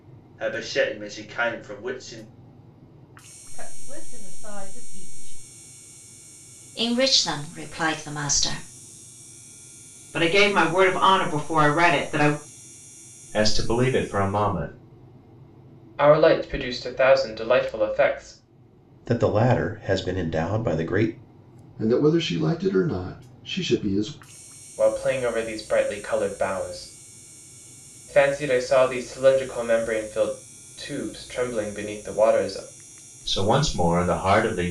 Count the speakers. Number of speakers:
8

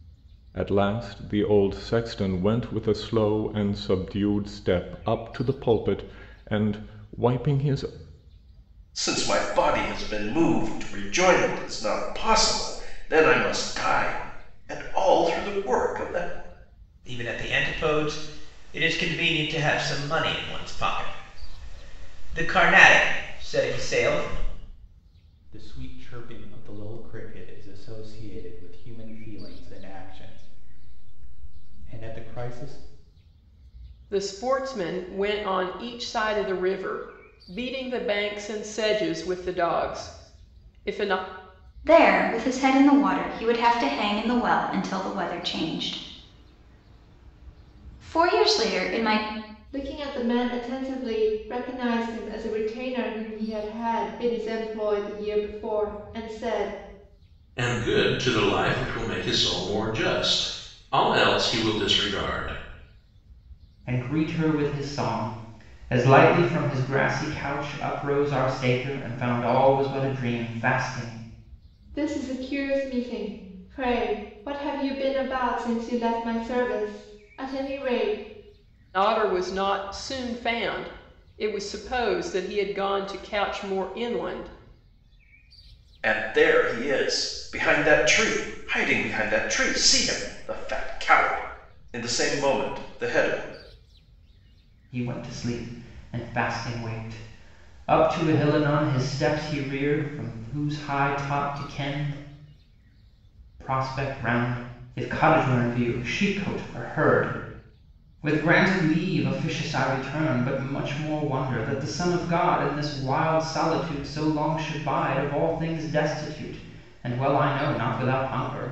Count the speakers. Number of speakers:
9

